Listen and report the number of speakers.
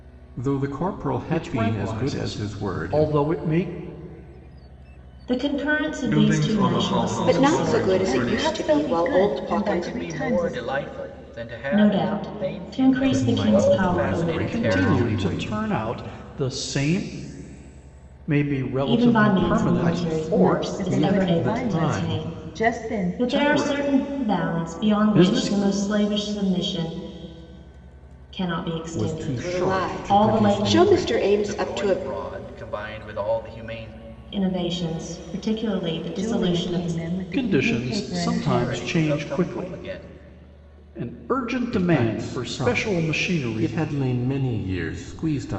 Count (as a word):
seven